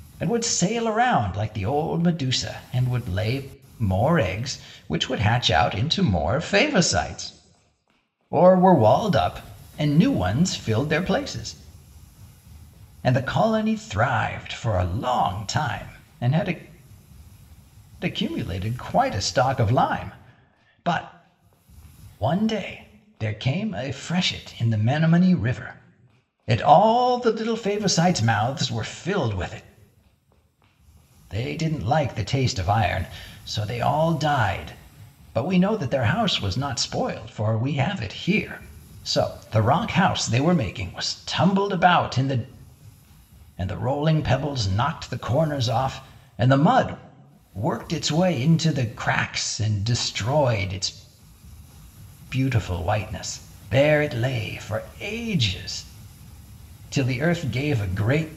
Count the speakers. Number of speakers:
1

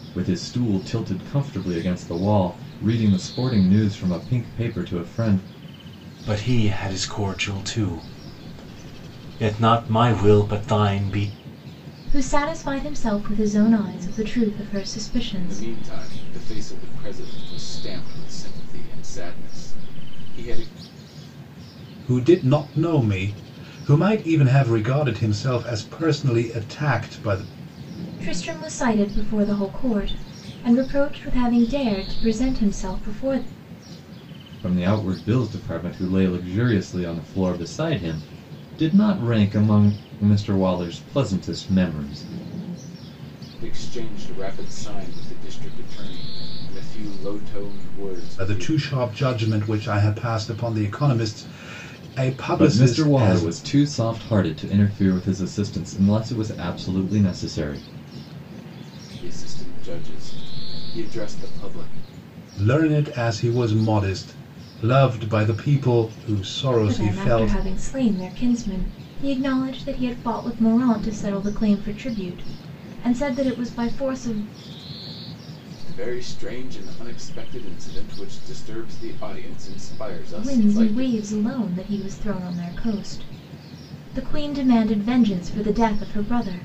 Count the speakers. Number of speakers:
5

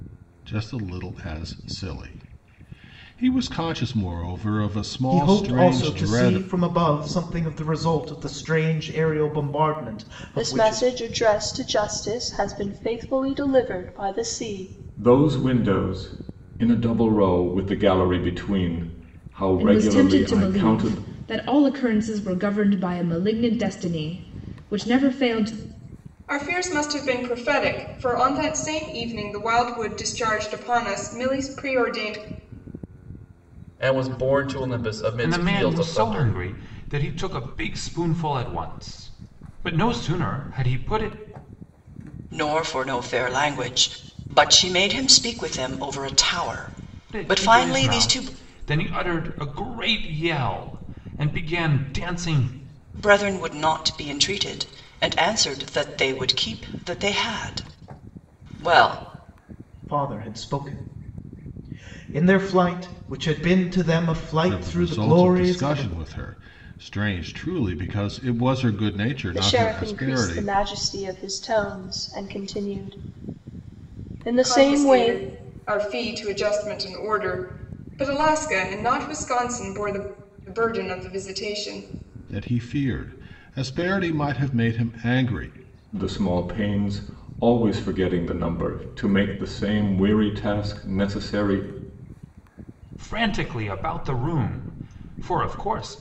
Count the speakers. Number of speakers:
9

